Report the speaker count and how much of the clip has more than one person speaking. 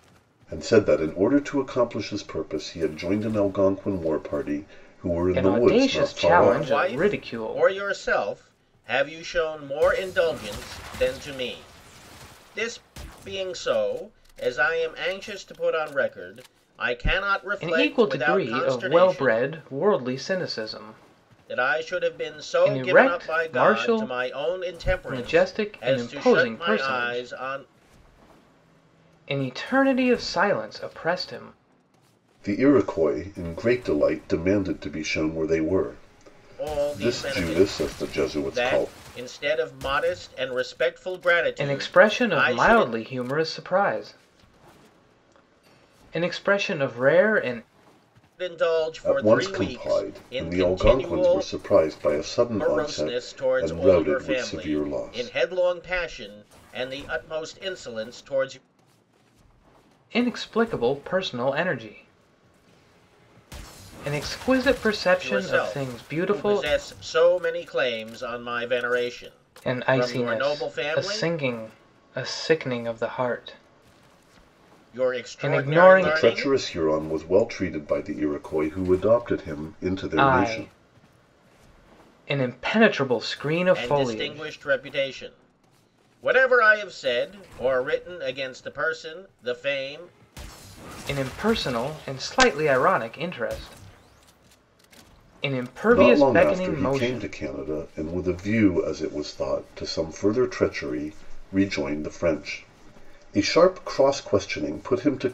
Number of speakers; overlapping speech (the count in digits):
3, about 25%